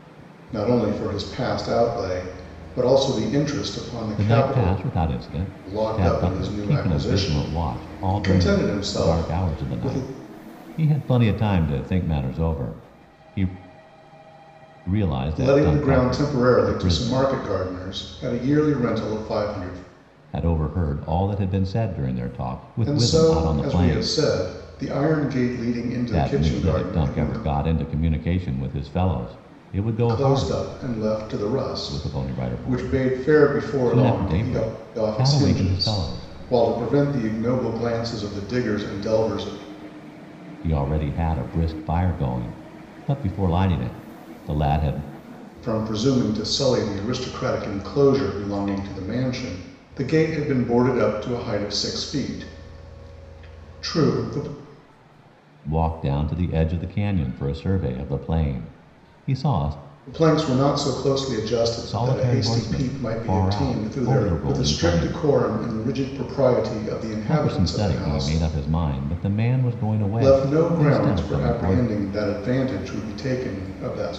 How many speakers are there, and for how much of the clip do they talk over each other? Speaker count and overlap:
two, about 27%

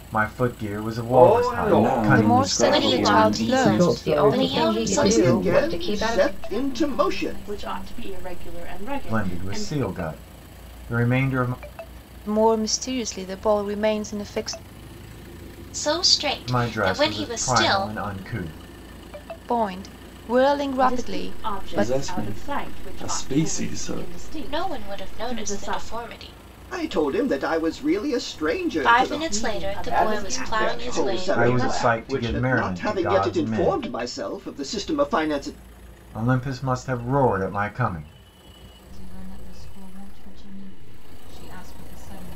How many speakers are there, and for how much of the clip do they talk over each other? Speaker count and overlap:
ten, about 45%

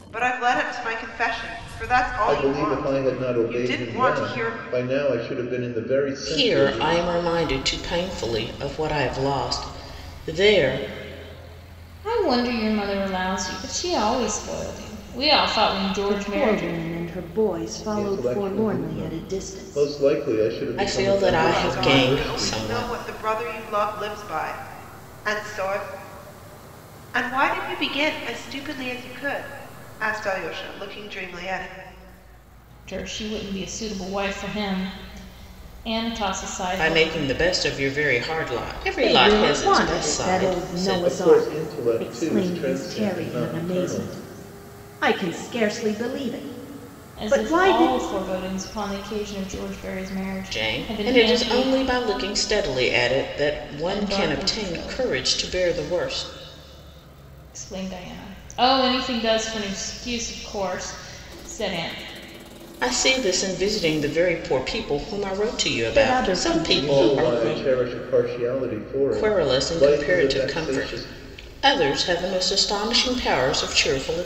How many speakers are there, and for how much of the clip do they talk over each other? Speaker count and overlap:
five, about 28%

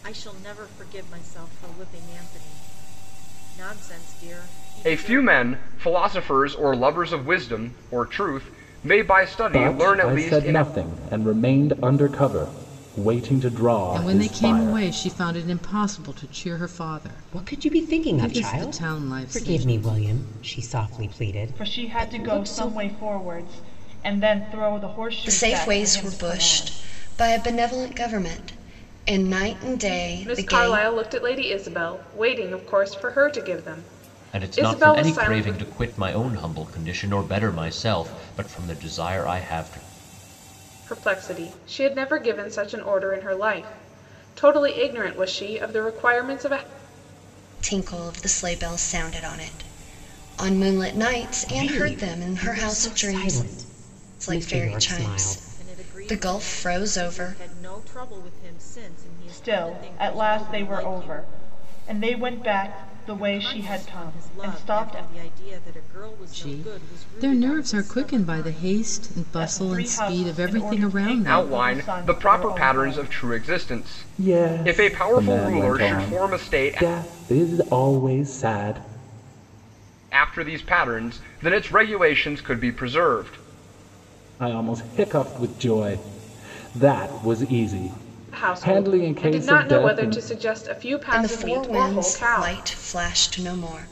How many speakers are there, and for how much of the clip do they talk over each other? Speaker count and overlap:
nine, about 34%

